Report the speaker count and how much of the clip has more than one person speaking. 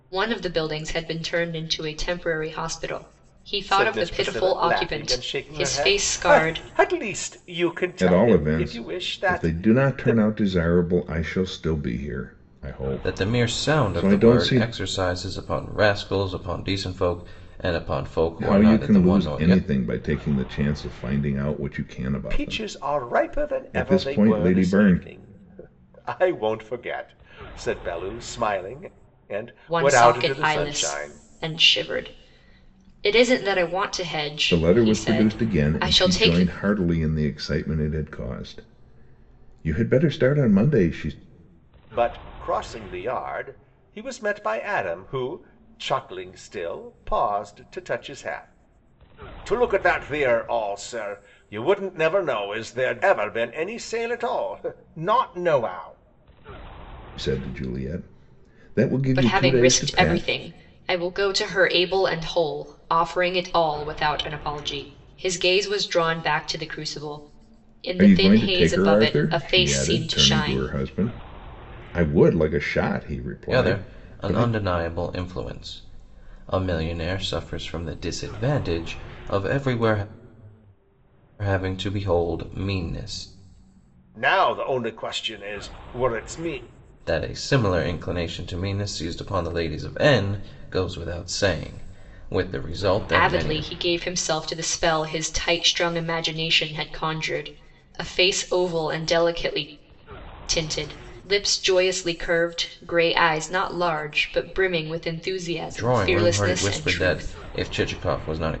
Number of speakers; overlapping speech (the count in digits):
4, about 20%